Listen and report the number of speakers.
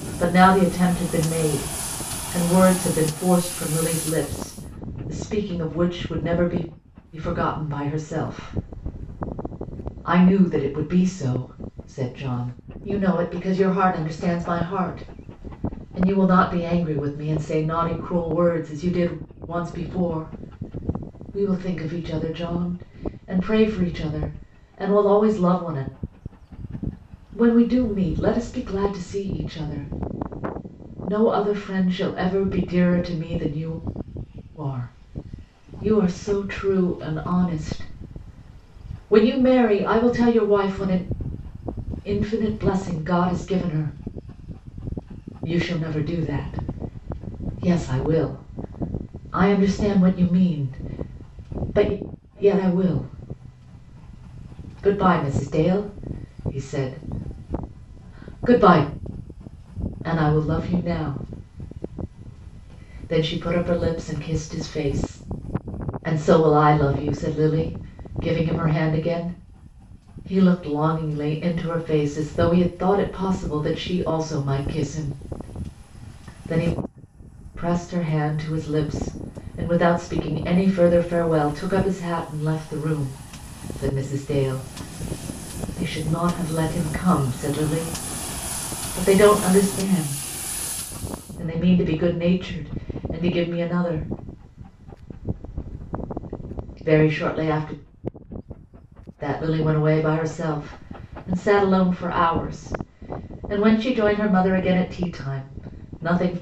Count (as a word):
one